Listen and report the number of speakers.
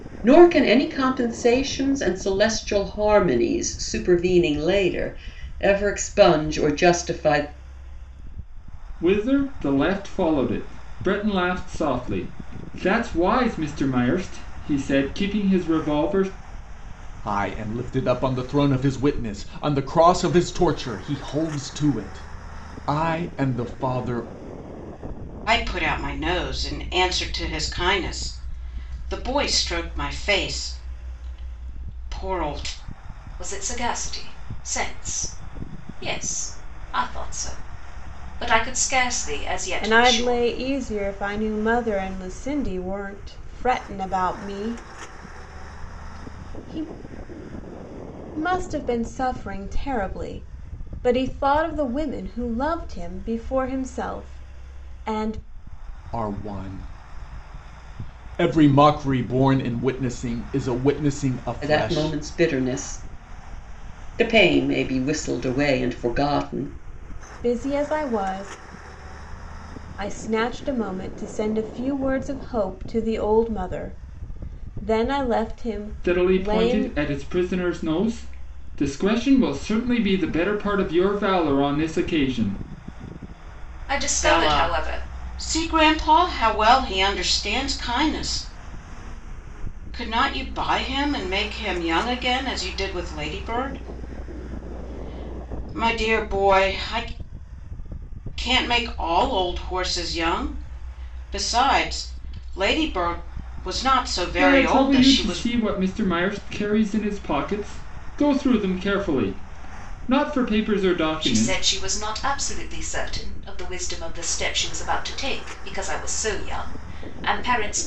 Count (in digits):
6